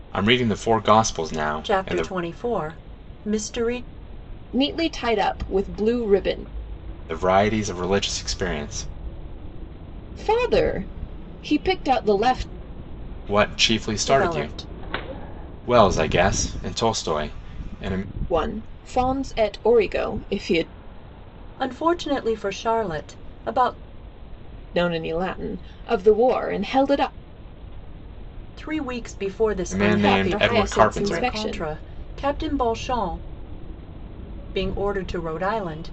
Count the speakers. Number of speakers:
three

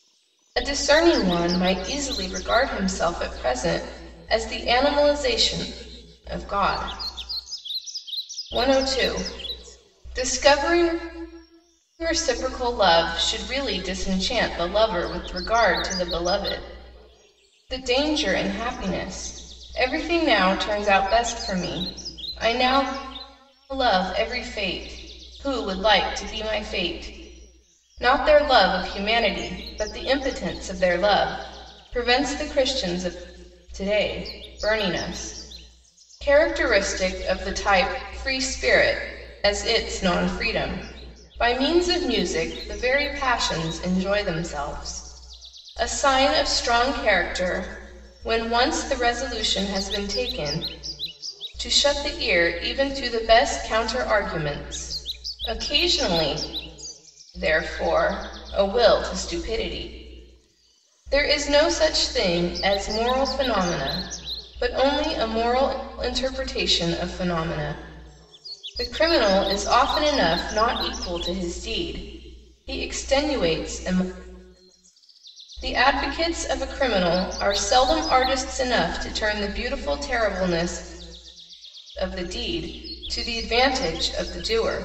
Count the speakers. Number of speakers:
one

